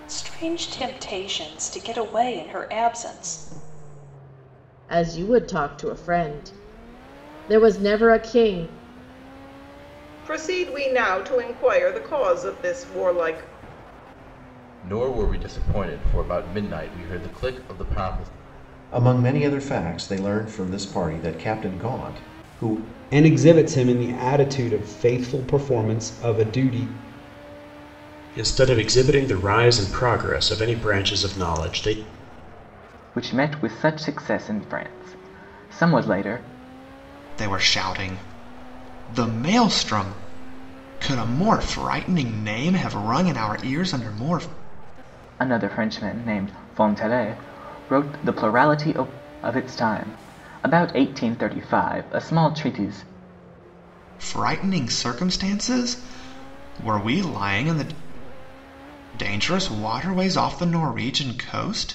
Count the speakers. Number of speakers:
9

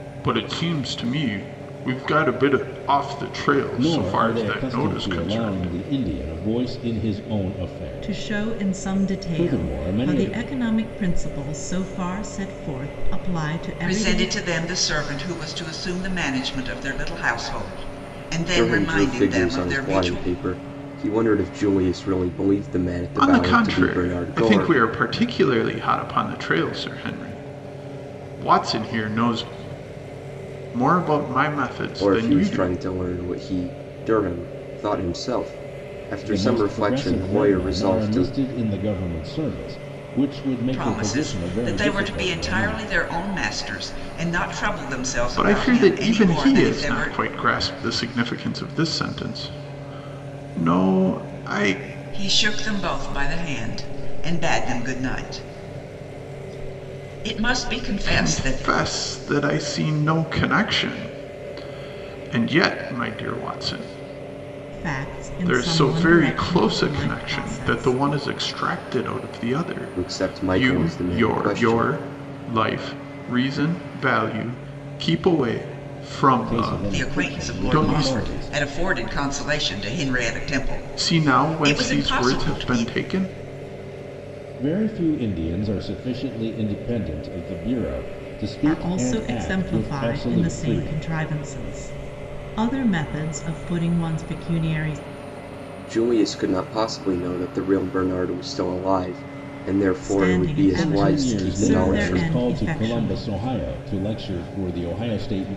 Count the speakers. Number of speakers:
5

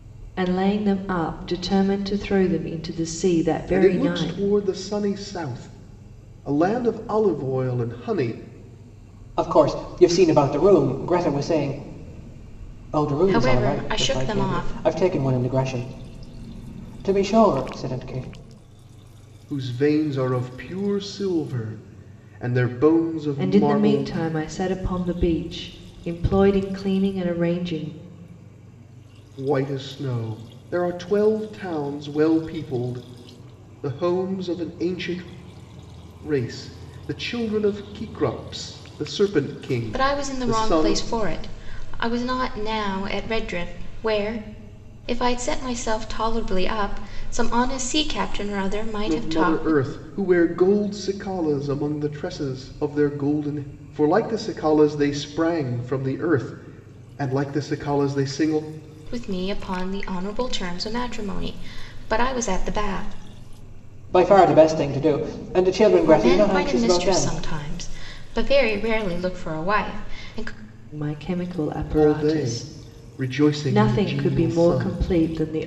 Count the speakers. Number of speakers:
4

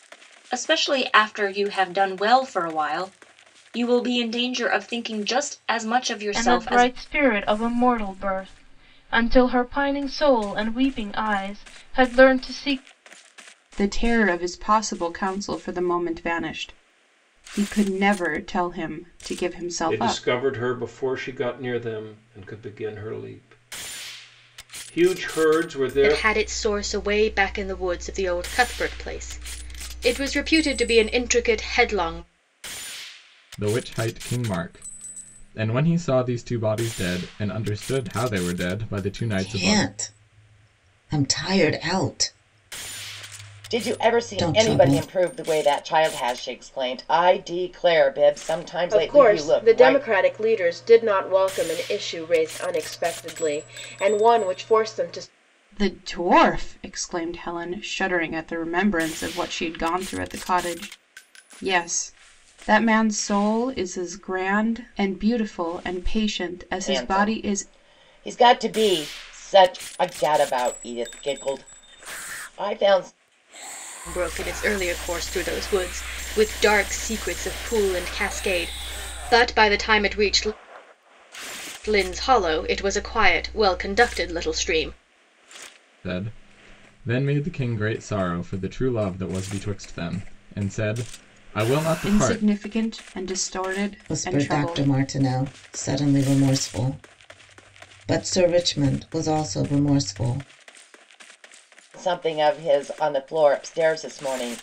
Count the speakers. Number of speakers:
9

